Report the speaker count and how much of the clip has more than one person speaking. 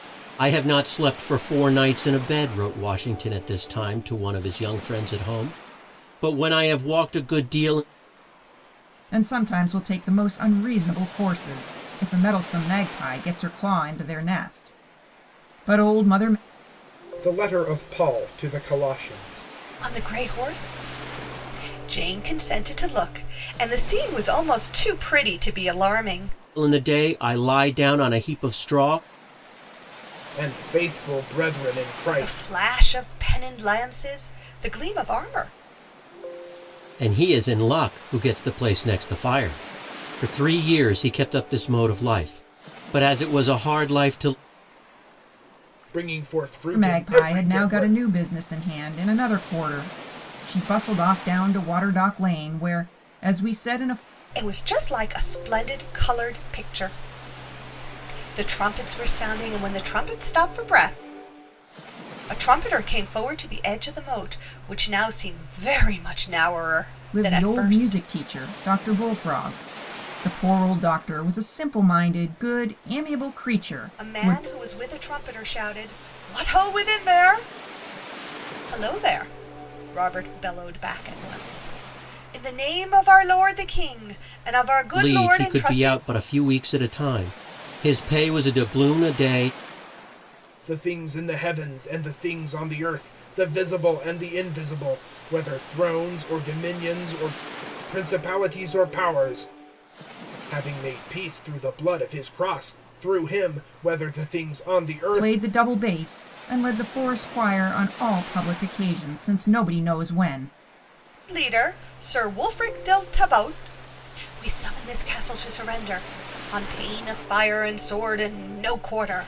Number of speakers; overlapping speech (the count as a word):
four, about 4%